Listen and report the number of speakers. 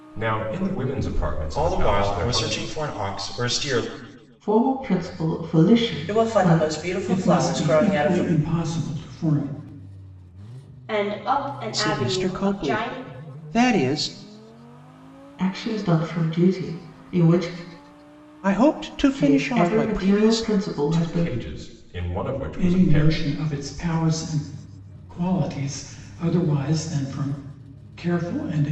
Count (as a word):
seven